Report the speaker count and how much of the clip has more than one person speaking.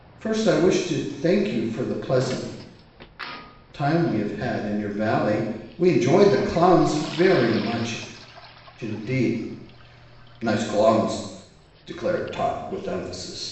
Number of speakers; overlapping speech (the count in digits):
1, no overlap